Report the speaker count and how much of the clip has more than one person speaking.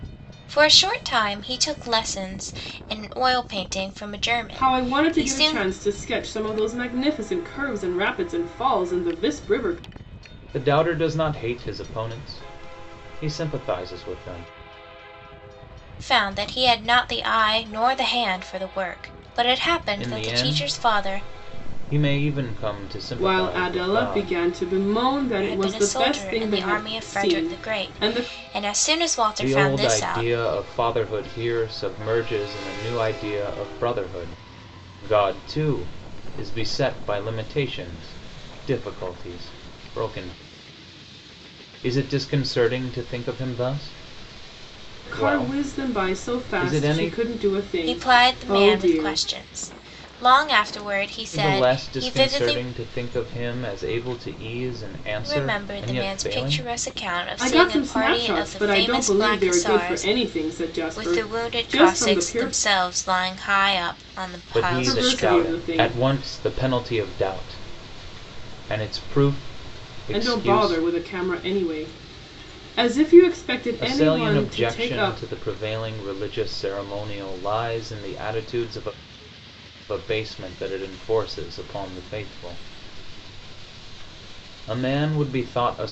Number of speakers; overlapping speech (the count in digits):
3, about 26%